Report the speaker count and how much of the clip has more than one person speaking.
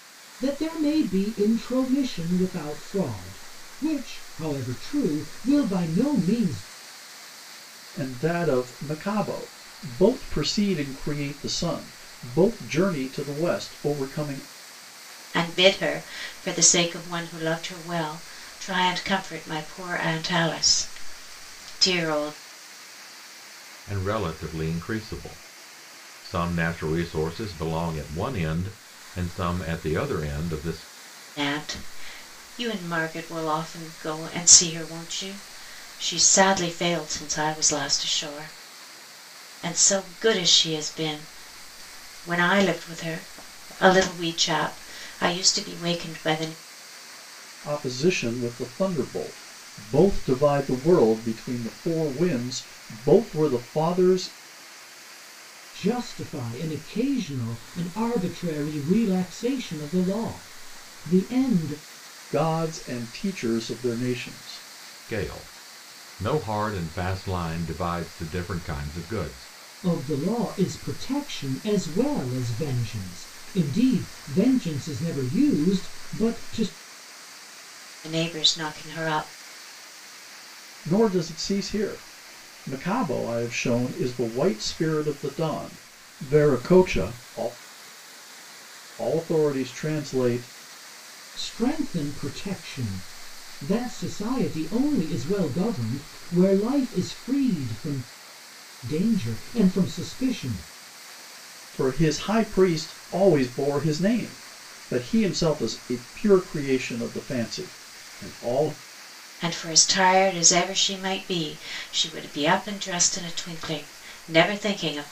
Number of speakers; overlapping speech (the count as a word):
four, no overlap